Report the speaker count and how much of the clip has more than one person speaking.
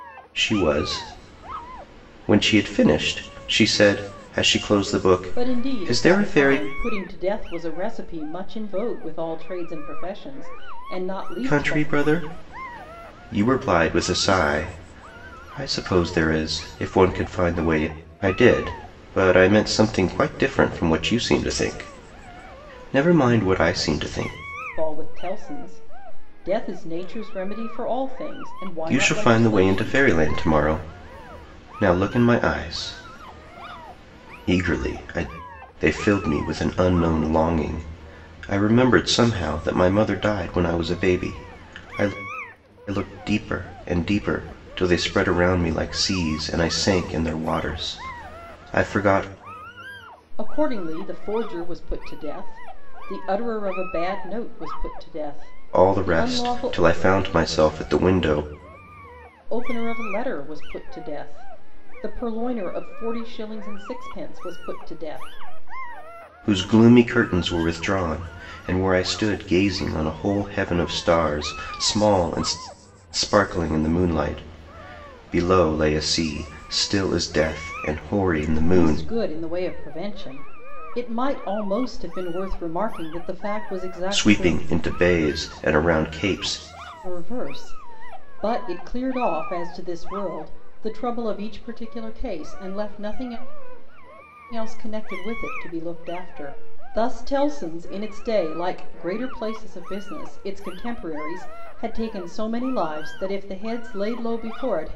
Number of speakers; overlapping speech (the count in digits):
2, about 5%